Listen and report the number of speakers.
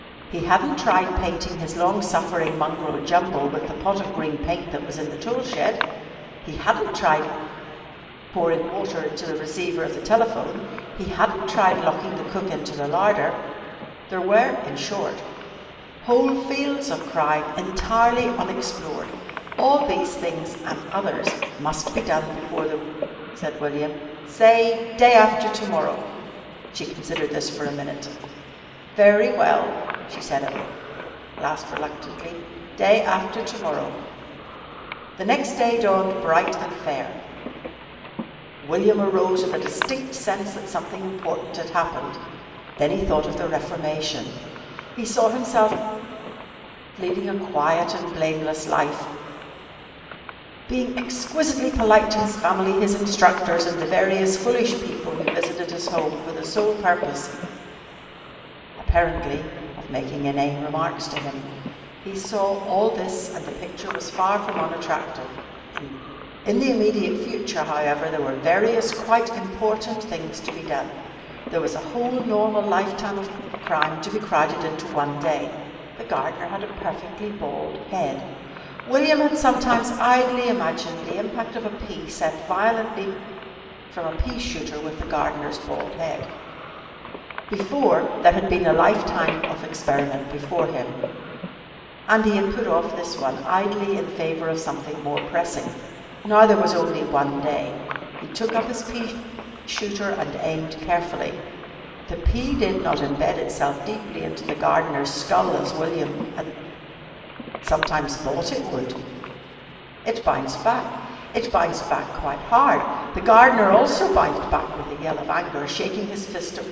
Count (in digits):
1